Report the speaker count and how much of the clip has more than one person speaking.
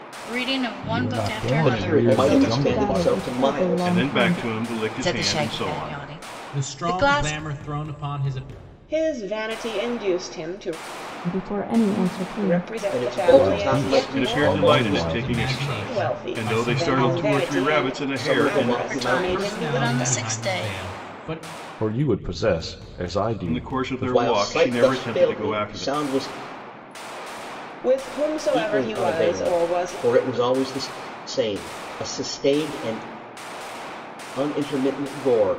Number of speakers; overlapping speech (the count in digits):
8, about 50%